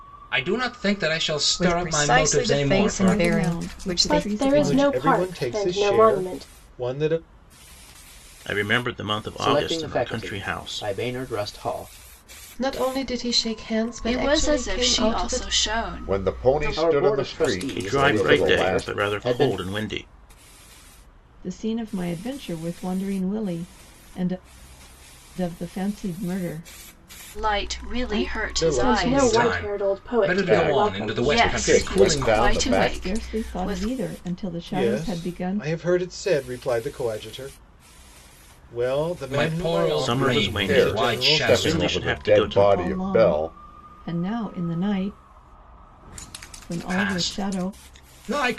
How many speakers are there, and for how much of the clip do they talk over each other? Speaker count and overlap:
10, about 49%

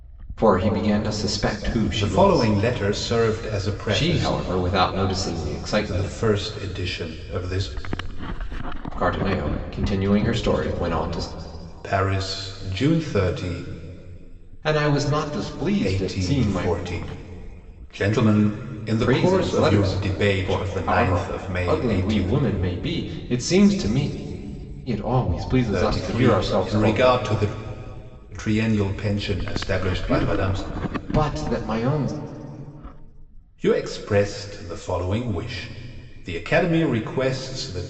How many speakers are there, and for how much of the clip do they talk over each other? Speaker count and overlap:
2, about 20%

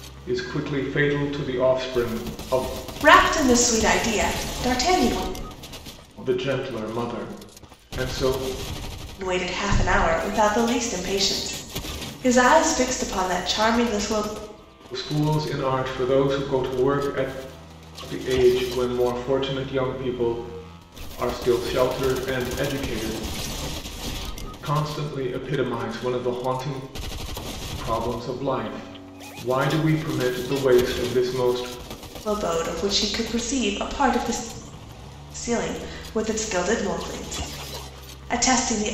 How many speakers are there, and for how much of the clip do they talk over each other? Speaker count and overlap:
2, no overlap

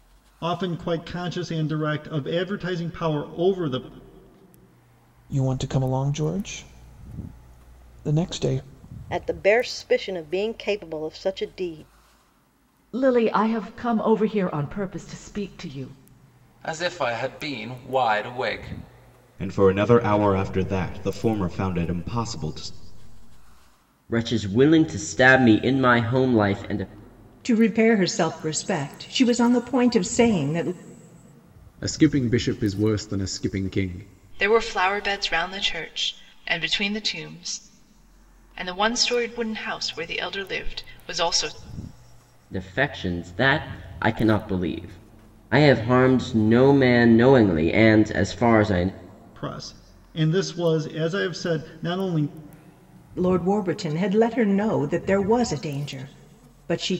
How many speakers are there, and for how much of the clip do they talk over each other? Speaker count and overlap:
10, no overlap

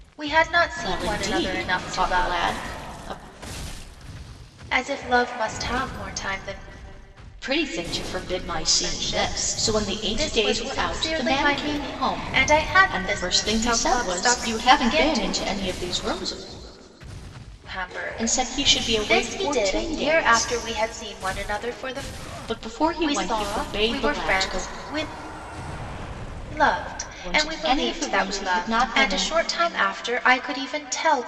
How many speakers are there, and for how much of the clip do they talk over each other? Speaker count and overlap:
2, about 46%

